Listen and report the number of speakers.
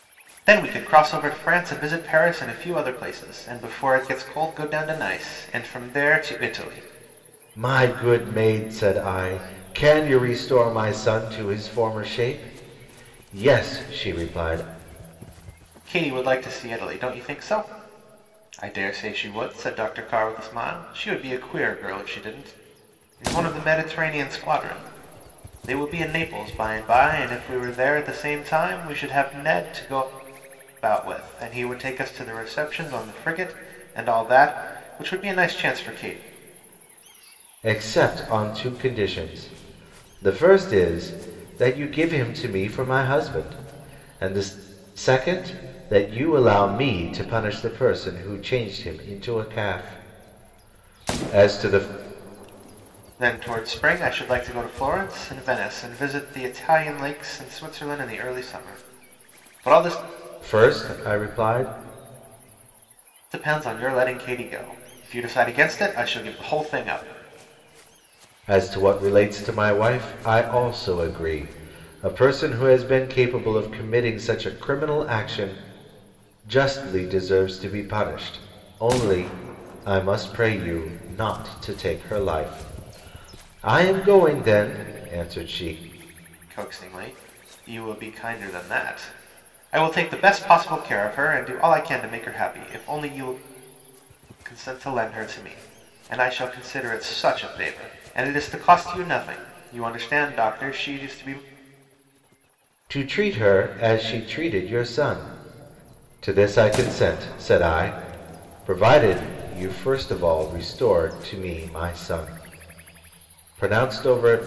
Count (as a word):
two